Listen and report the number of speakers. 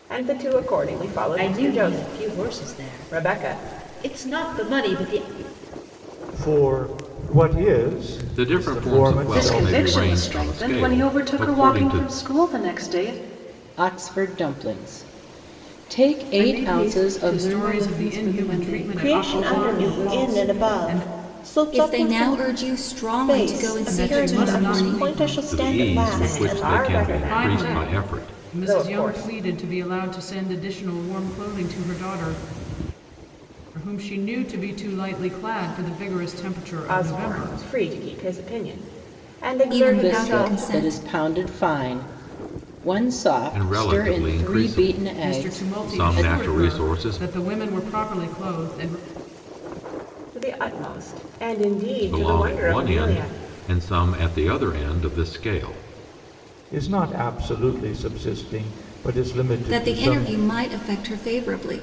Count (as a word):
ten